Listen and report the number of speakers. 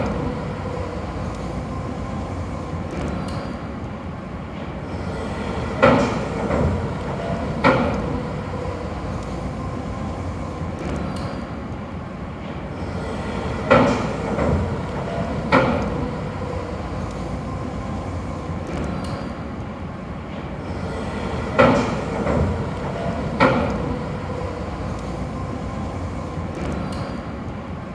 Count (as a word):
zero